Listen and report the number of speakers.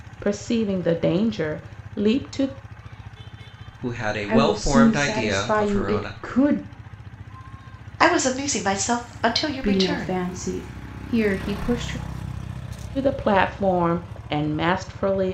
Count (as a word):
four